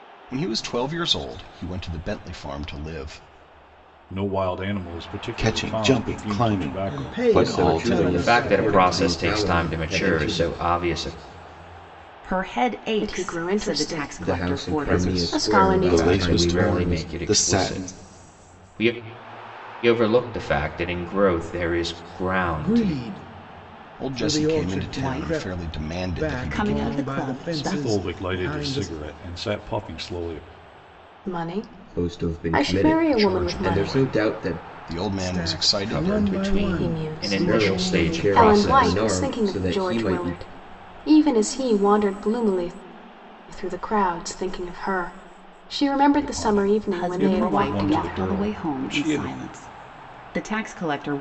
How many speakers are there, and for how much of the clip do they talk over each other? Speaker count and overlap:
8, about 53%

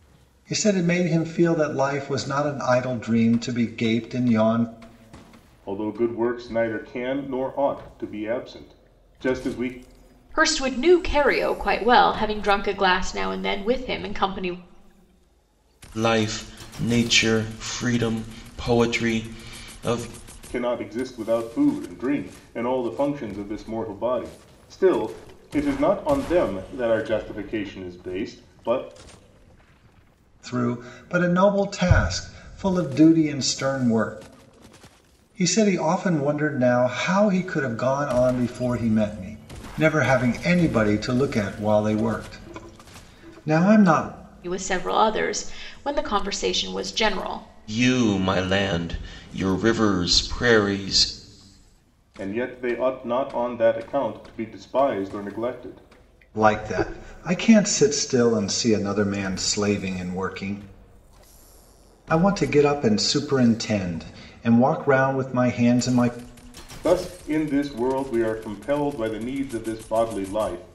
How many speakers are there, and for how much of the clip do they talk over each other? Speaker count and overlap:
4, no overlap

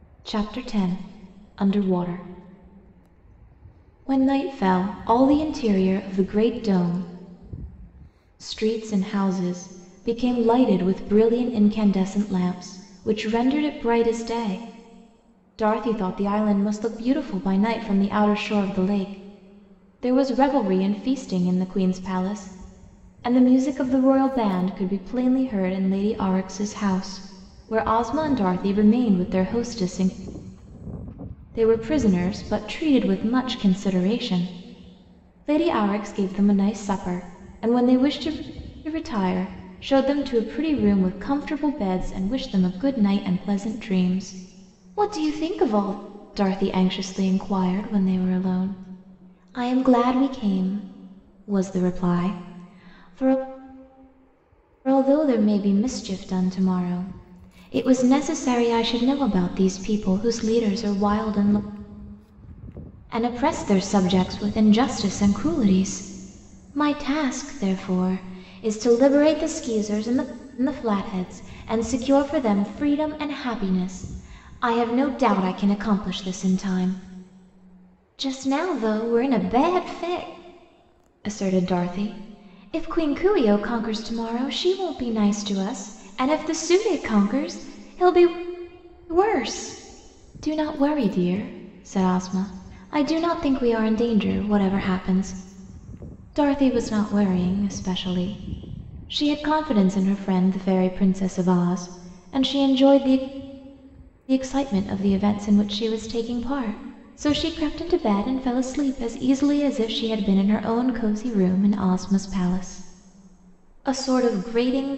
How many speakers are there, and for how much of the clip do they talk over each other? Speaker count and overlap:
1, no overlap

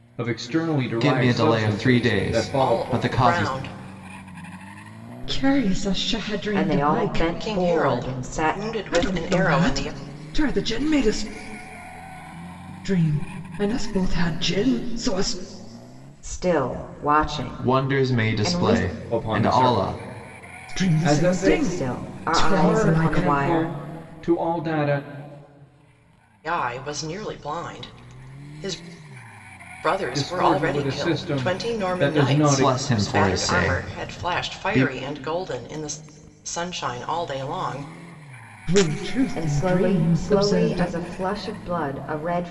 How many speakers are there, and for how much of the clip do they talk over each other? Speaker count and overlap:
5, about 41%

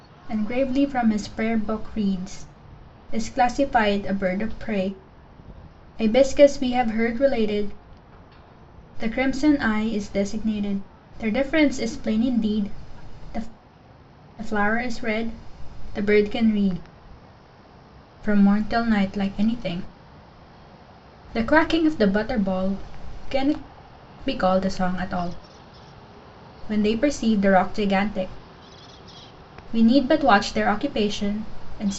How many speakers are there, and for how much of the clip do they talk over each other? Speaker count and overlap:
1, no overlap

